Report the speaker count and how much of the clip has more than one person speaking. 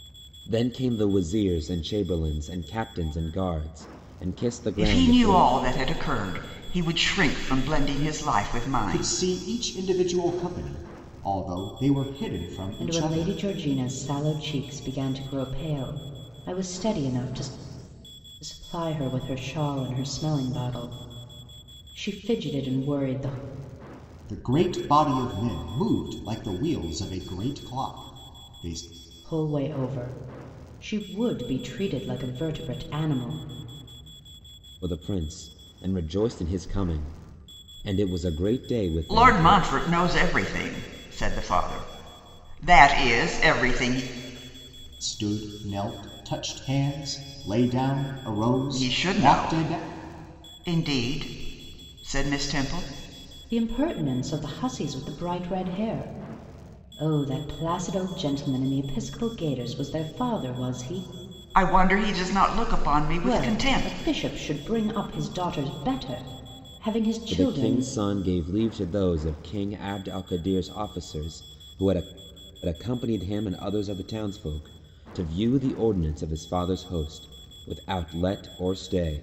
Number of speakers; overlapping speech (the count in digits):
4, about 6%